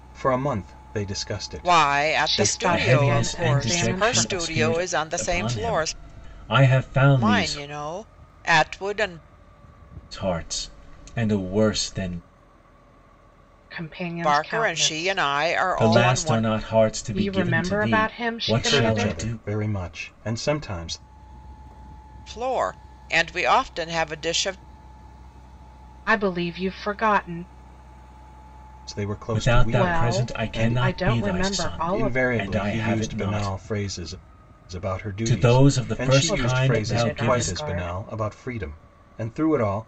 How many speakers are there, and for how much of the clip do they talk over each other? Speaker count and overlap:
four, about 40%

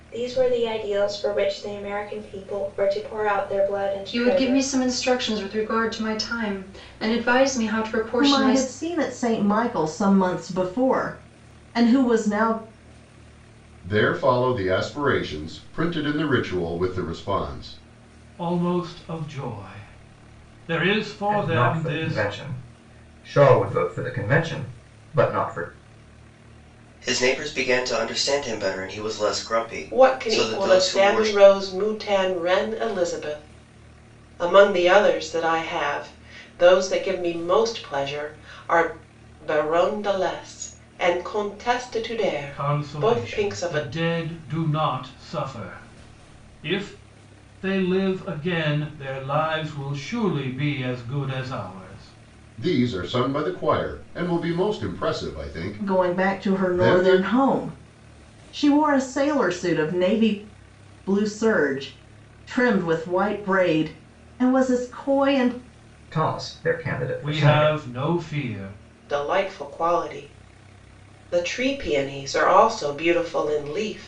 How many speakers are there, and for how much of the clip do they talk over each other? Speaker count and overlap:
eight, about 10%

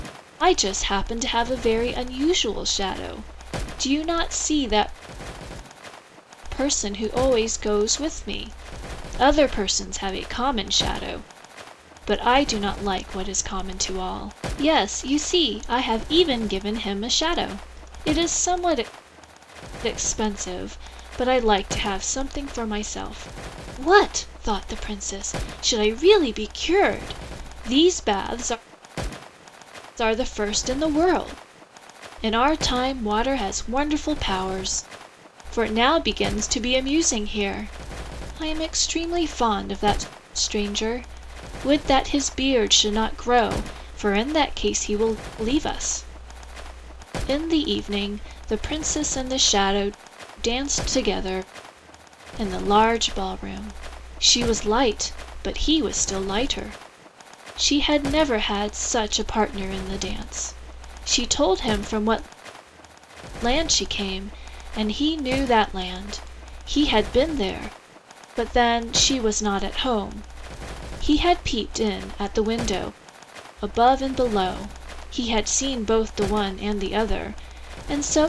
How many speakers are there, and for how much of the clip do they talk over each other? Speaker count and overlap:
one, no overlap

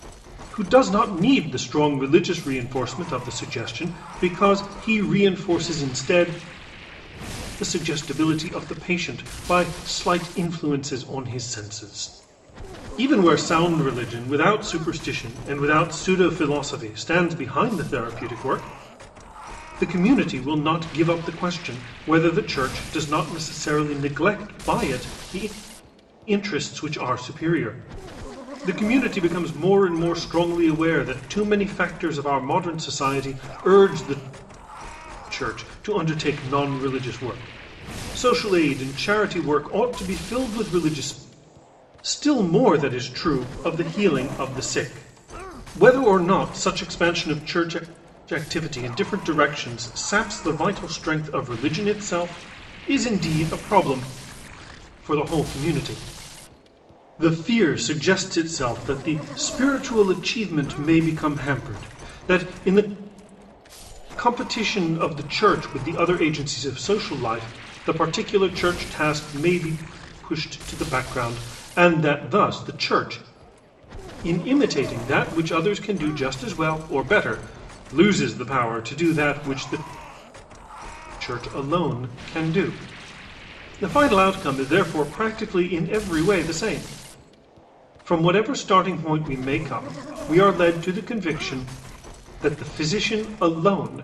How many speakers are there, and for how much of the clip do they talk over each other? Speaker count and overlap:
one, no overlap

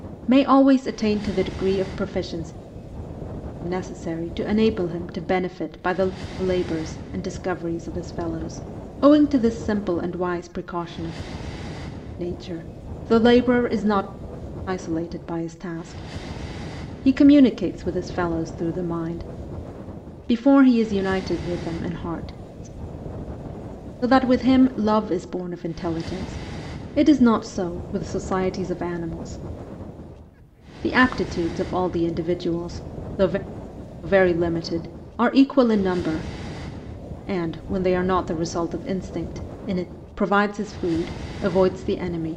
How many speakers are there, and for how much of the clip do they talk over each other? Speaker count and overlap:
one, no overlap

